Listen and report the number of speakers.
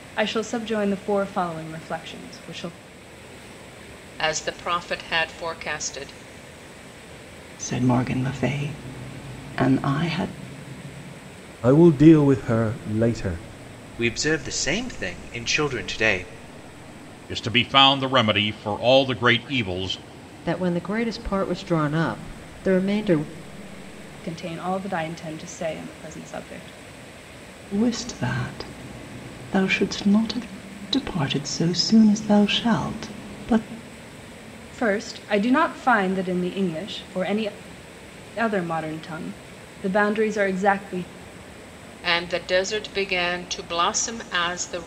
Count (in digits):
7